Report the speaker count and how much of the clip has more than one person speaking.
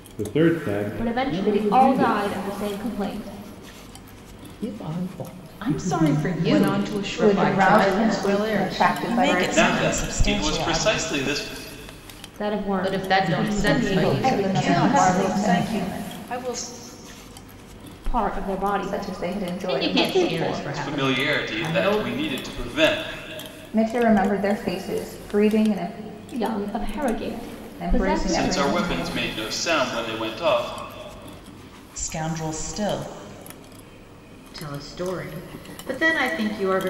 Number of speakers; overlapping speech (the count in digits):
9, about 43%